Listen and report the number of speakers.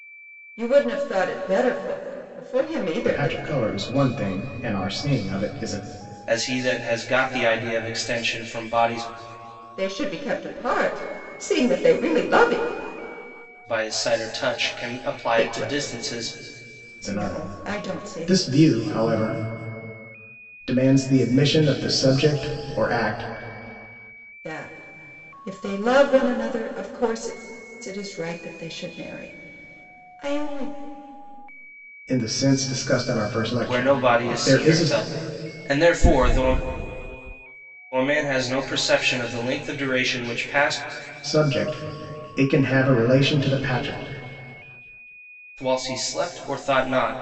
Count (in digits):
3